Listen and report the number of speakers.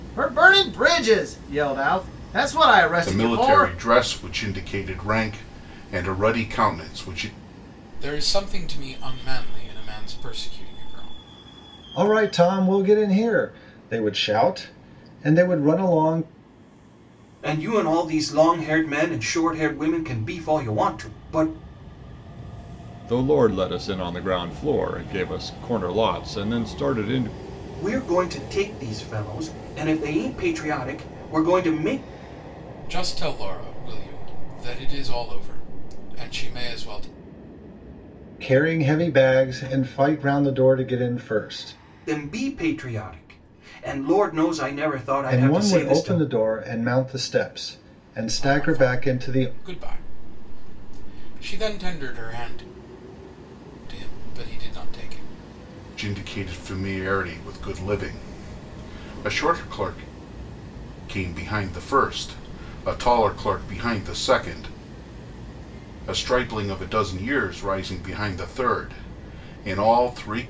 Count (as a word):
six